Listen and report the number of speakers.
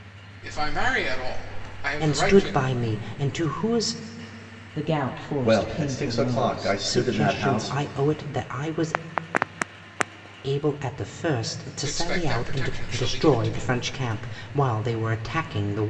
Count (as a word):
four